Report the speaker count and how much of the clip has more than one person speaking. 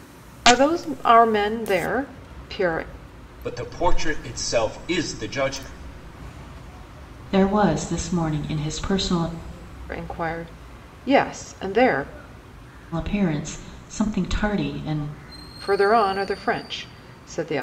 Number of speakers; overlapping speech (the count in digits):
3, no overlap